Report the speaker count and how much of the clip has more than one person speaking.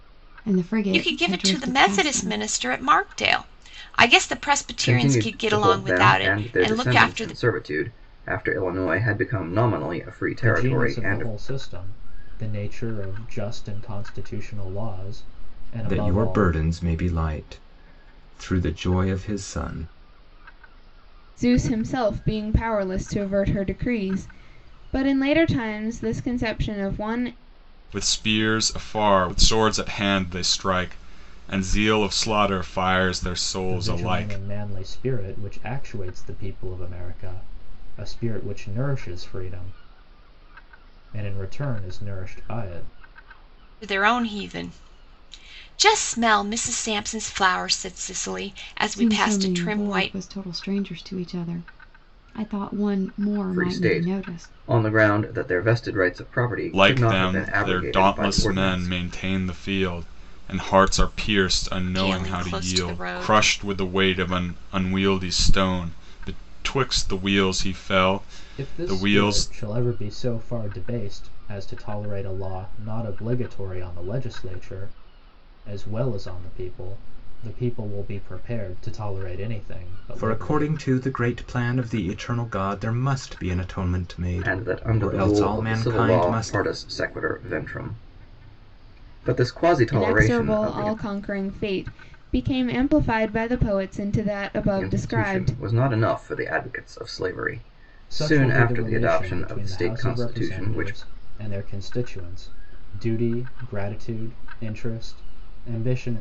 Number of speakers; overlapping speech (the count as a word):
seven, about 20%